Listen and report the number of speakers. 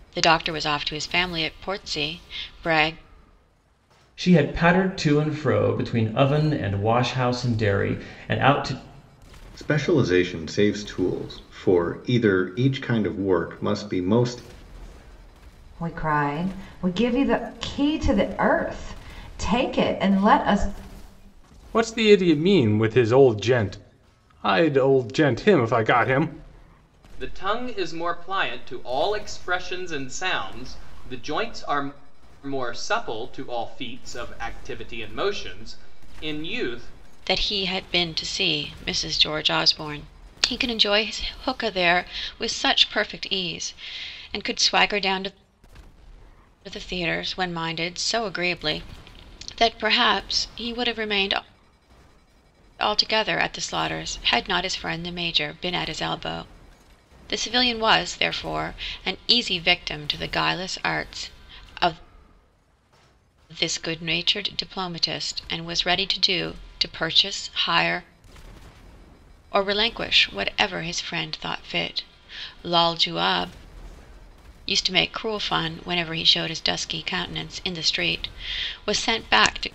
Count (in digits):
6